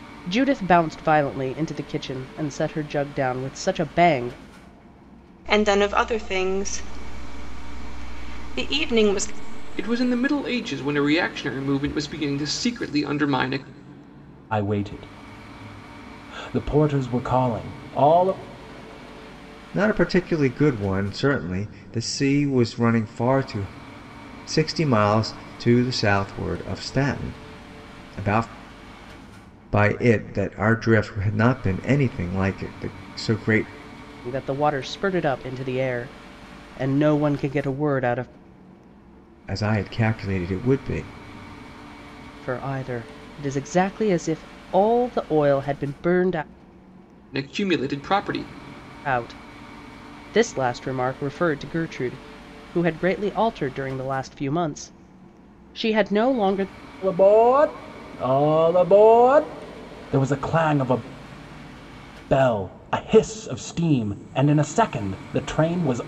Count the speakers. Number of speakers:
5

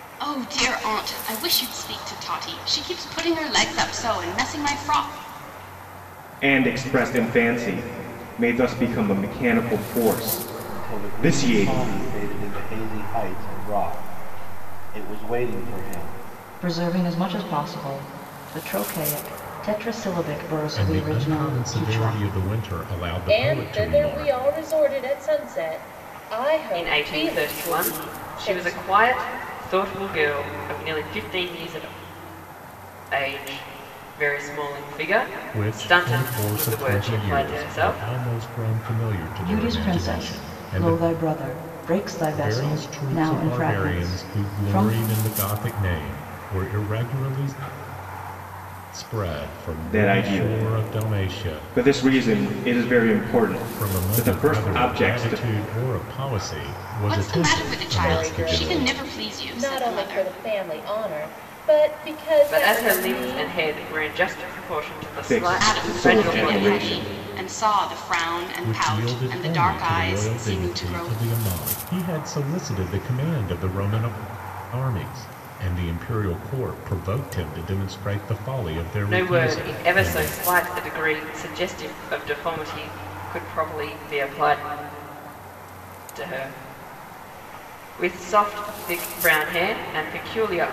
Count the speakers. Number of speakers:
7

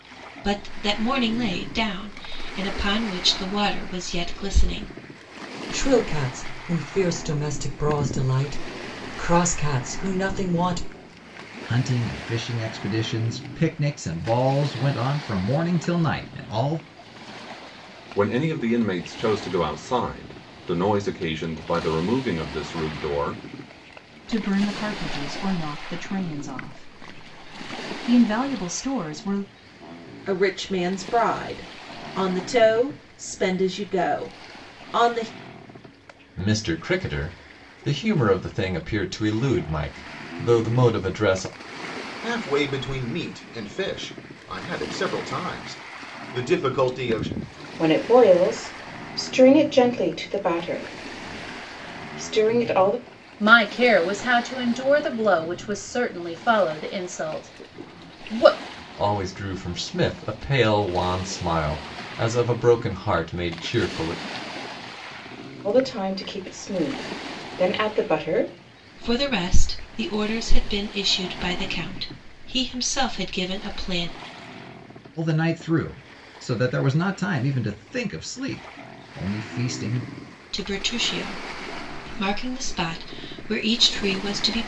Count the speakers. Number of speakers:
10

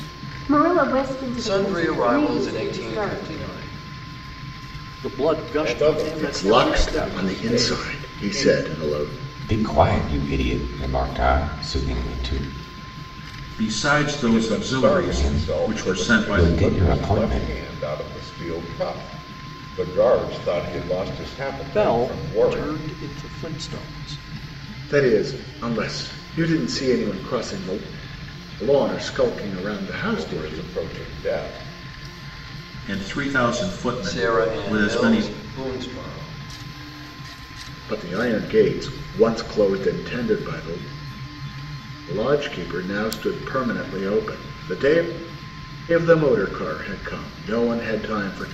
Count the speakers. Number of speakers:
7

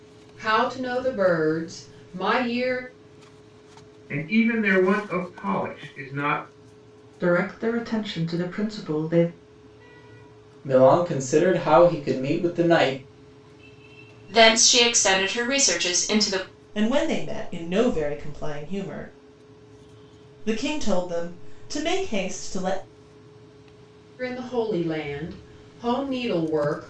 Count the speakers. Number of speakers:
6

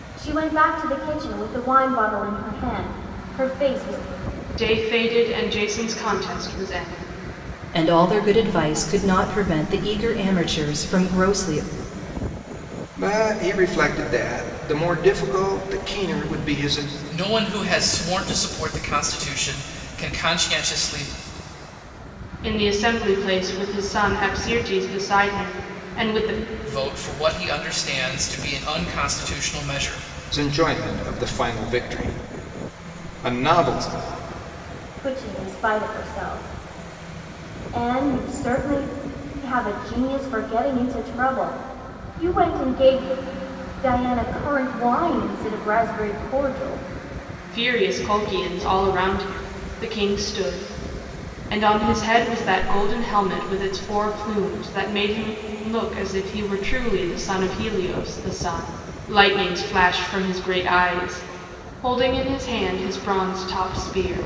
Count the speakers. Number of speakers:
5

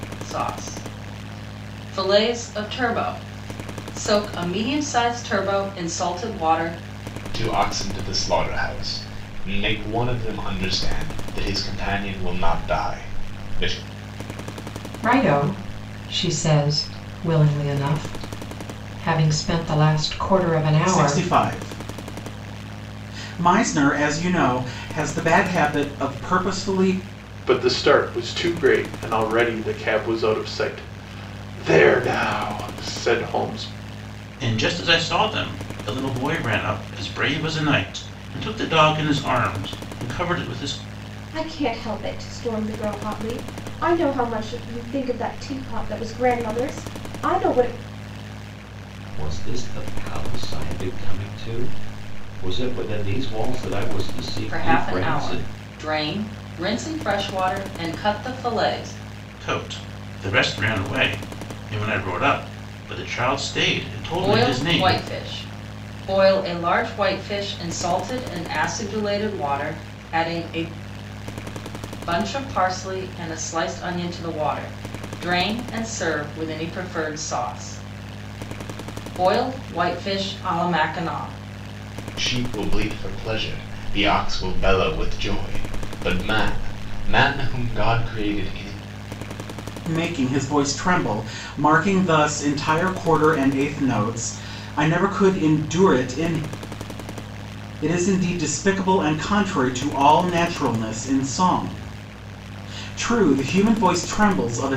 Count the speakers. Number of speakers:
8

